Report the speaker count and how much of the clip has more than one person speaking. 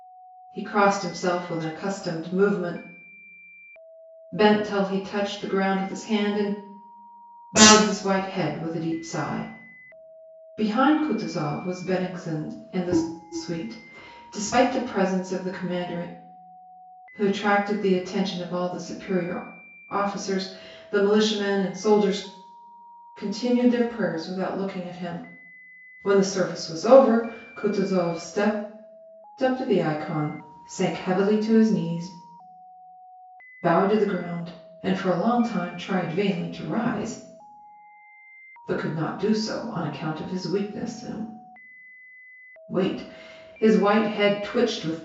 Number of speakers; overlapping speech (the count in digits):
1, no overlap